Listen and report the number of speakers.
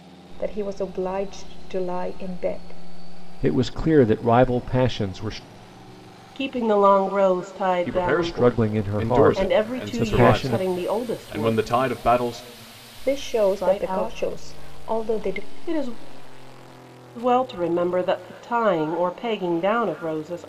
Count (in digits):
4